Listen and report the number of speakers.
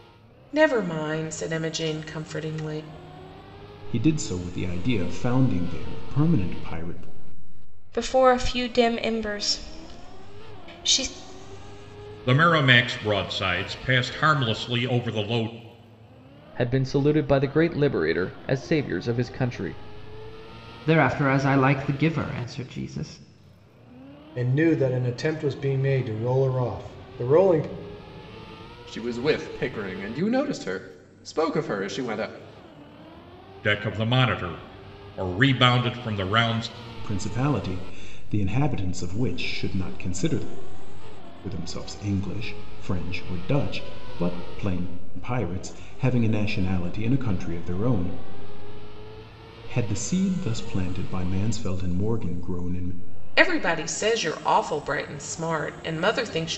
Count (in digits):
8